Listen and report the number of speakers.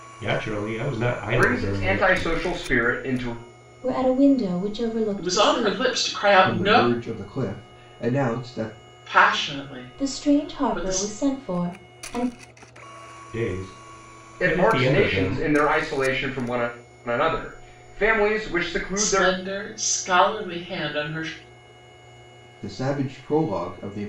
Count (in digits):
5